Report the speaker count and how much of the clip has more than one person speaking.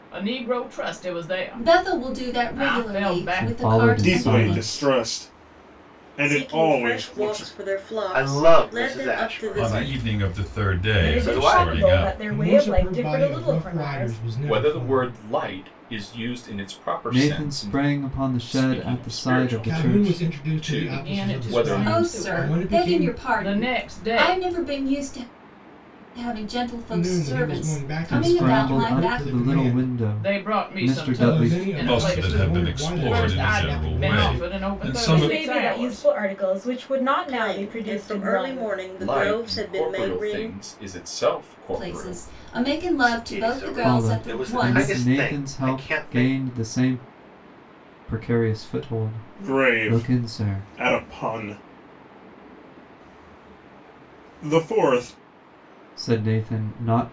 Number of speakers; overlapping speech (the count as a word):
ten, about 62%